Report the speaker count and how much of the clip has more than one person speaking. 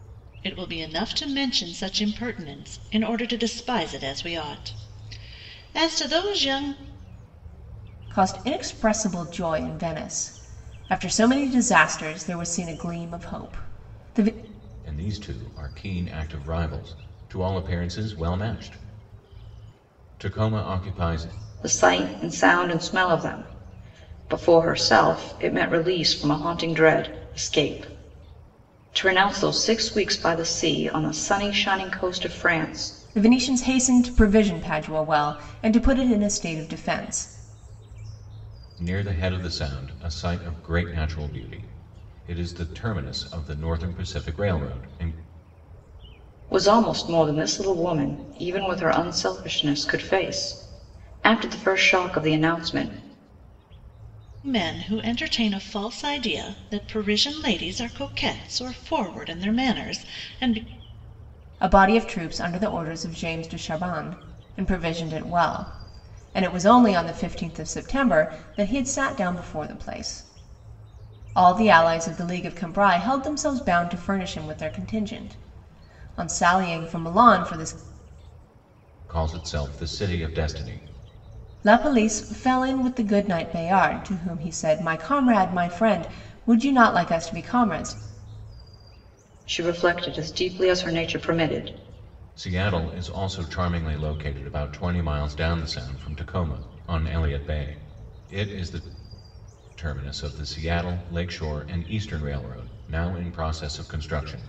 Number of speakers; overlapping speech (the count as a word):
four, no overlap